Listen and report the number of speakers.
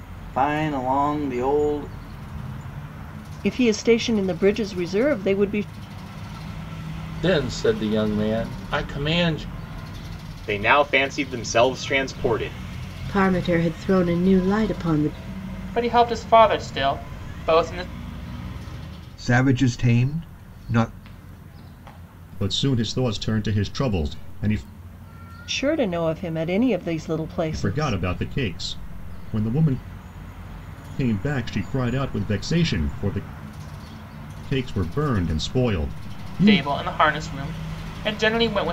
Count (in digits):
8